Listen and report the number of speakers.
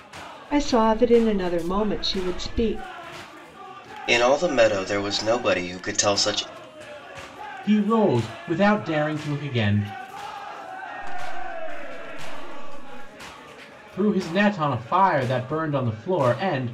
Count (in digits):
4